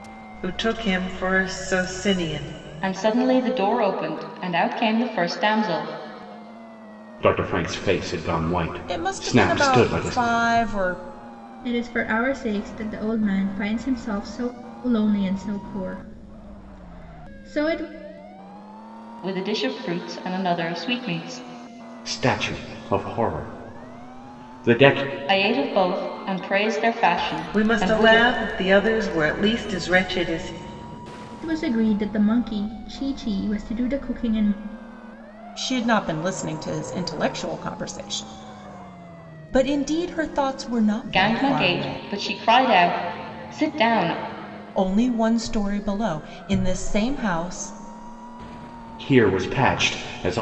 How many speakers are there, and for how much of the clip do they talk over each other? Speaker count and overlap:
5, about 6%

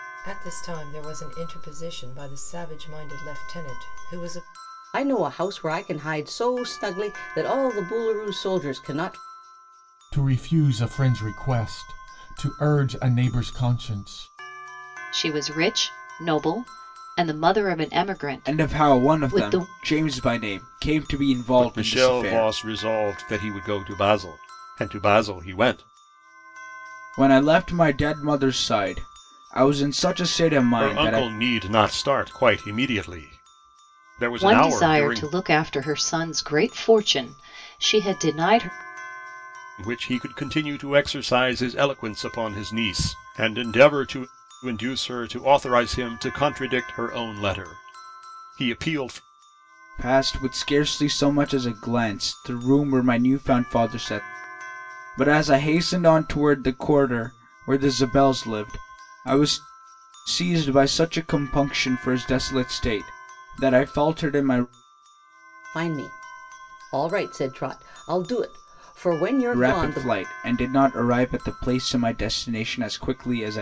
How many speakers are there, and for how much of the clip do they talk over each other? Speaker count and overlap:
6, about 6%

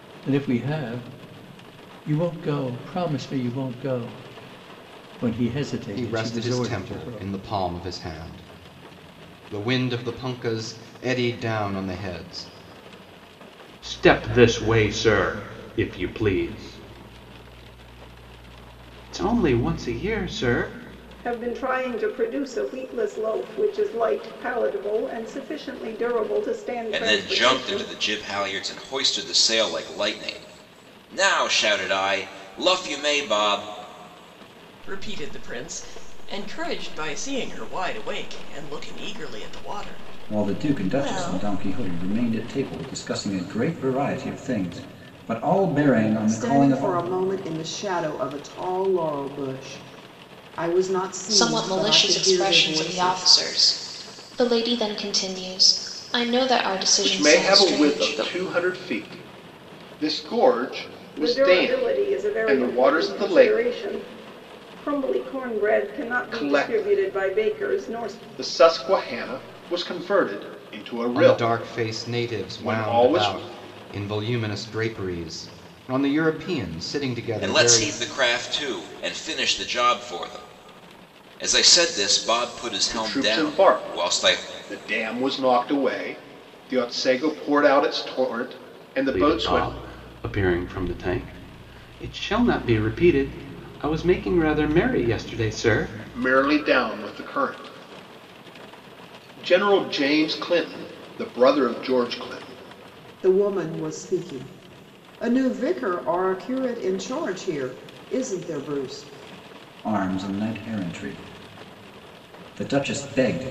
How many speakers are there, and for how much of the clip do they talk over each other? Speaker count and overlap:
10, about 15%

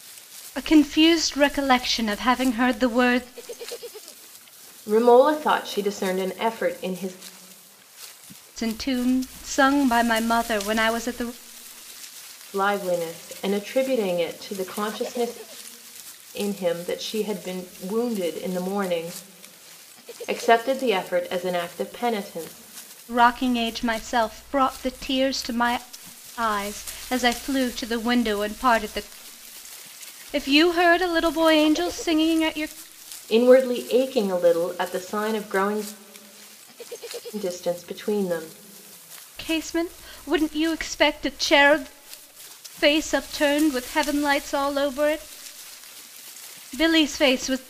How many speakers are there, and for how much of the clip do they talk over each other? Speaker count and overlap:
2, no overlap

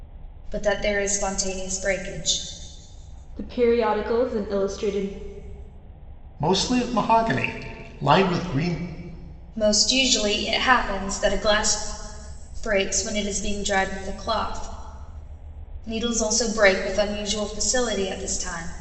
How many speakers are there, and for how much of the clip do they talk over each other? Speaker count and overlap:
3, no overlap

